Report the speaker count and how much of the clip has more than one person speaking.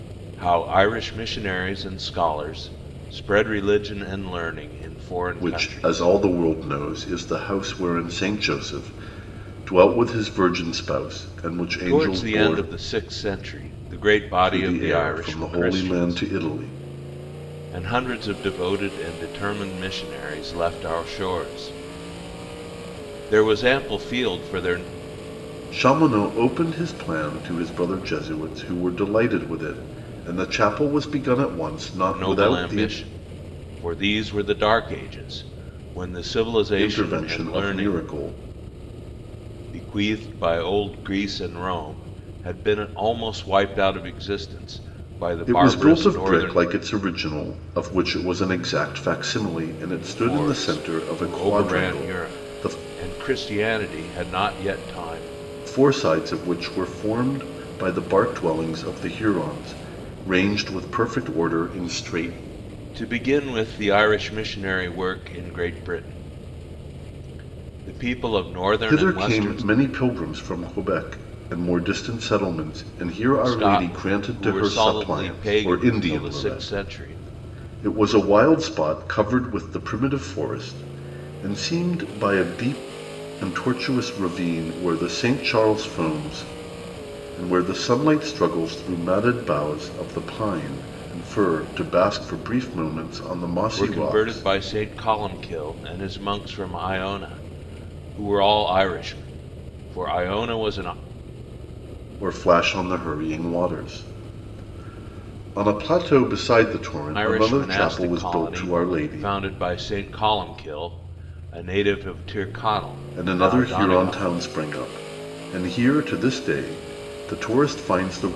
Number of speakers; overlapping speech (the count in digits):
2, about 15%